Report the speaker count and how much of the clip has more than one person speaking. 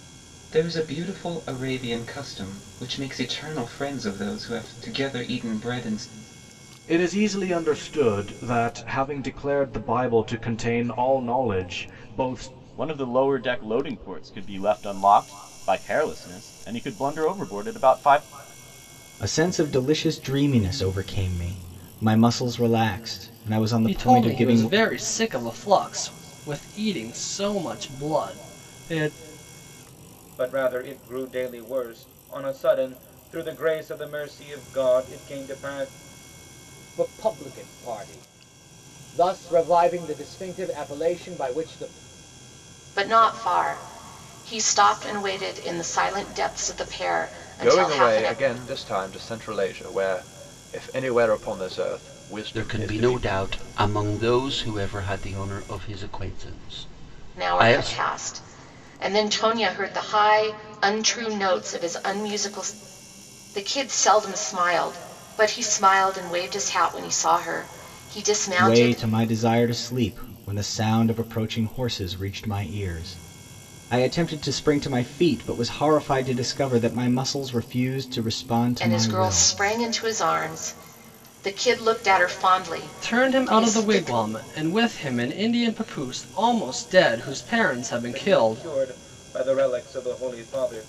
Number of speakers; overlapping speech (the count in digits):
10, about 7%